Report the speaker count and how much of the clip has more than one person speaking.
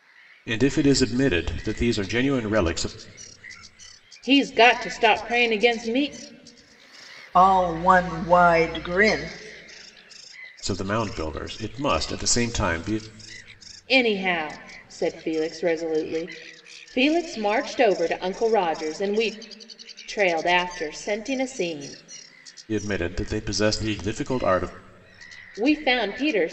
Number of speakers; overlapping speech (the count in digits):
3, no overlap